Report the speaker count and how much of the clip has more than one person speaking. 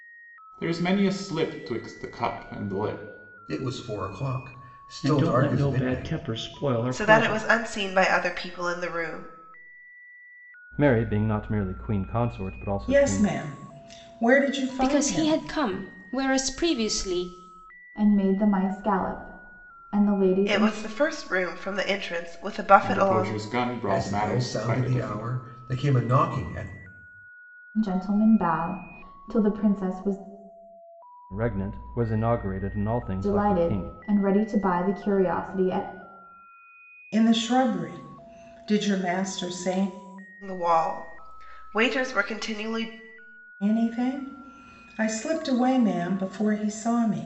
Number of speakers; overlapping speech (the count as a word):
eight, about 13%